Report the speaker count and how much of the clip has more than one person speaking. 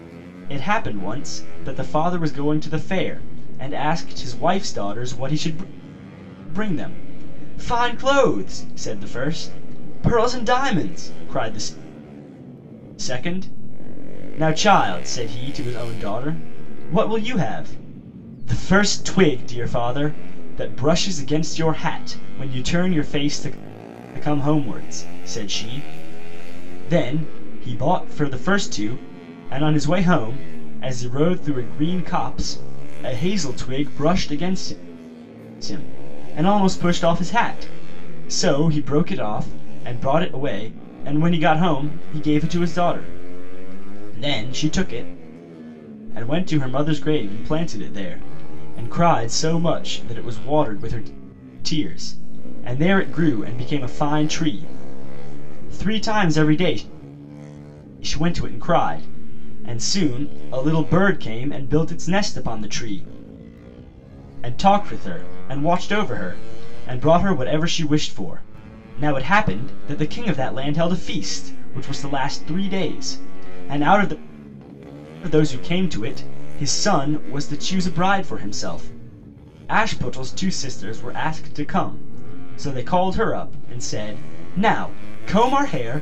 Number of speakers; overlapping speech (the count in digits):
1, no overlap